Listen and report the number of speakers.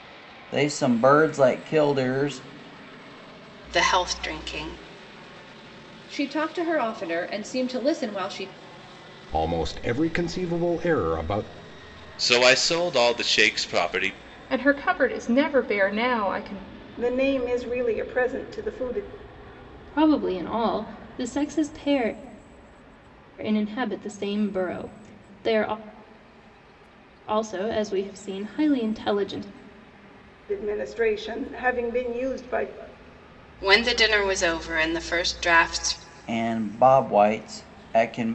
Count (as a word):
eight